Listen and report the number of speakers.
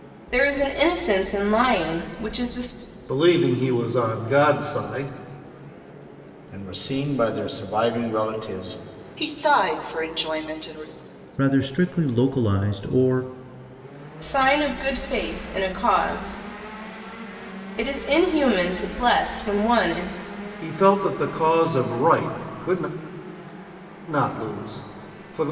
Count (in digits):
5